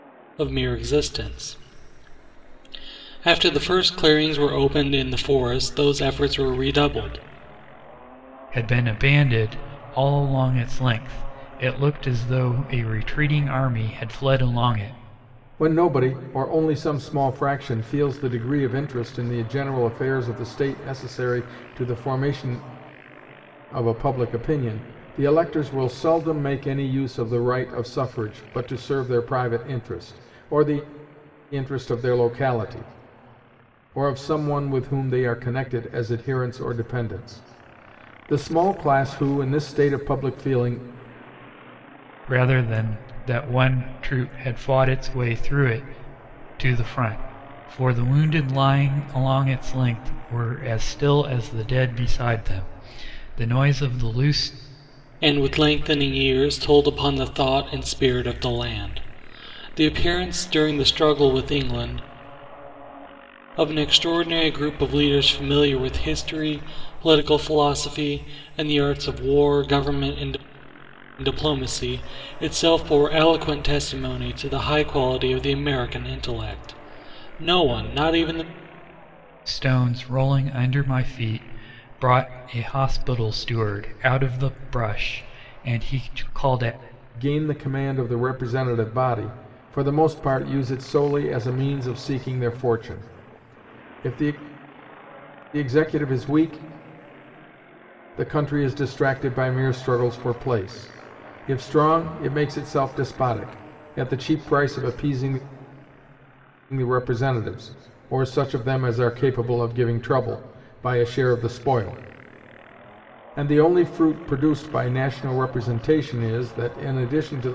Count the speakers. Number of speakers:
three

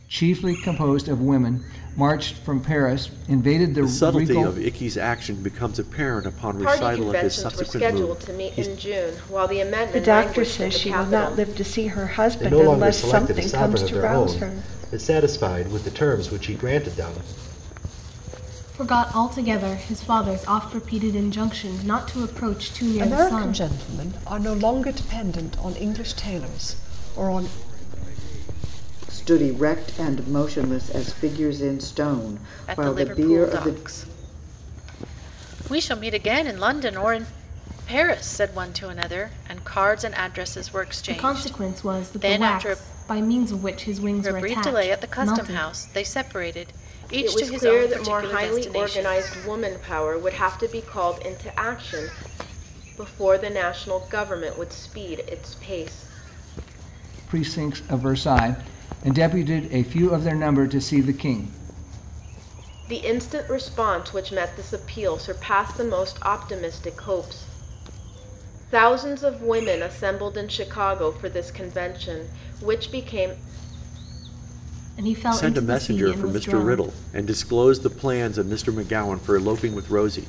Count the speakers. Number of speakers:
ten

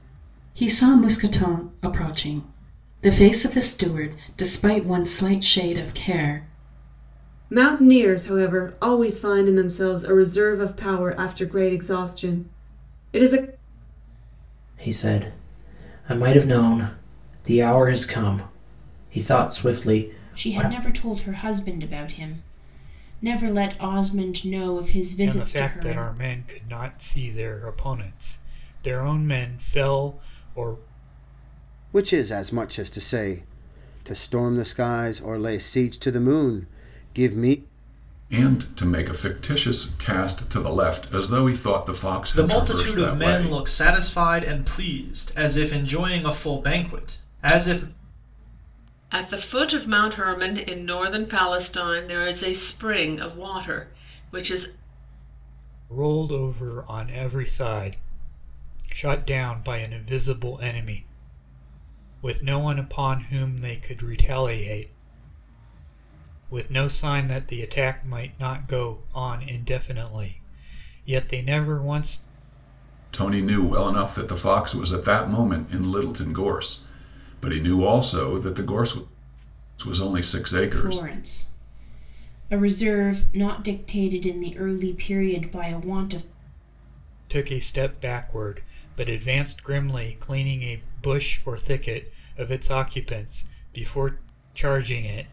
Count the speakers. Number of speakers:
nine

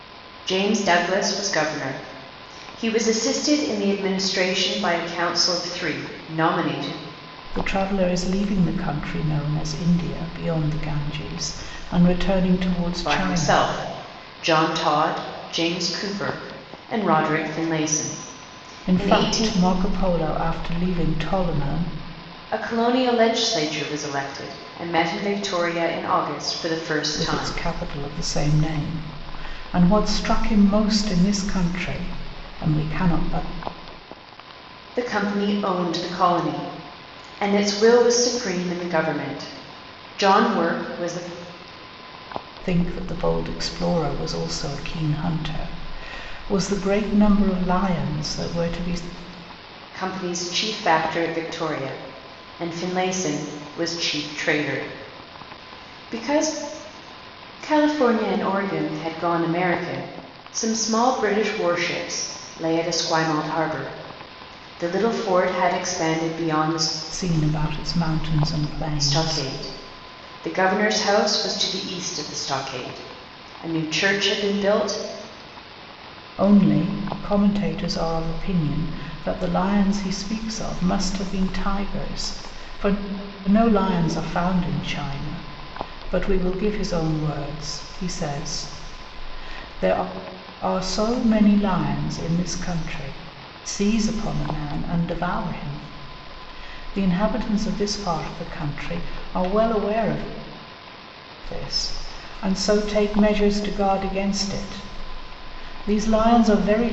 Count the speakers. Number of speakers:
two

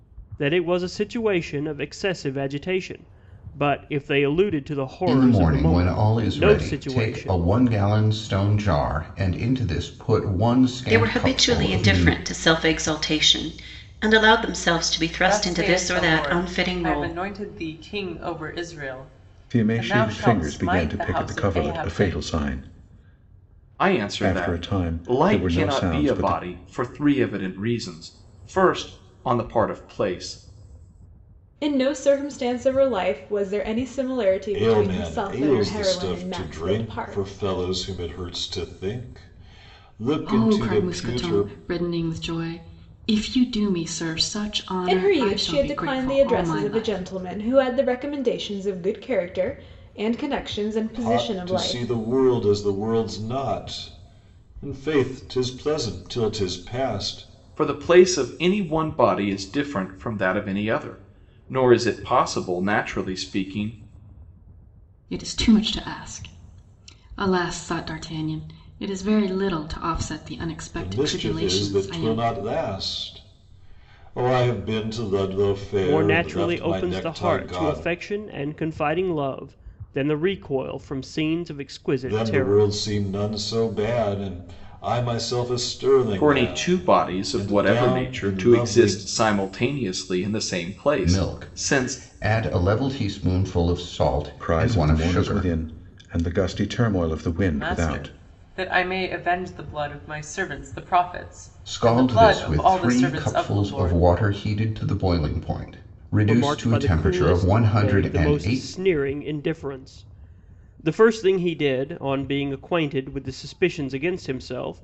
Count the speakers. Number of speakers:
nine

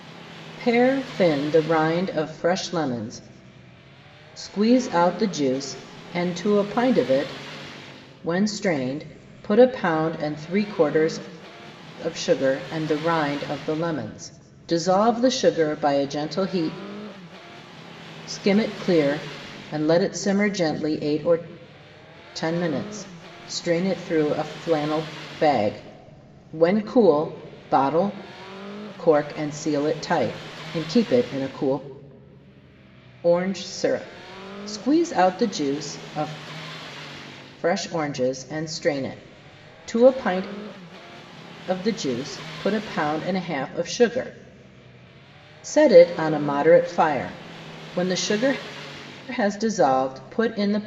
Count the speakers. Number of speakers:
one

